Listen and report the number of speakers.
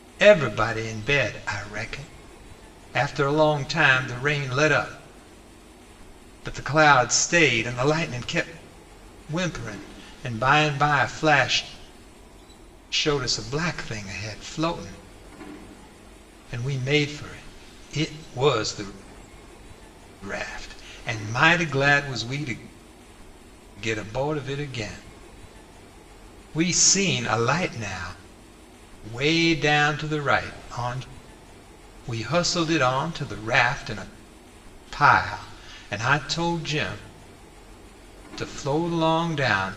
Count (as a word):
one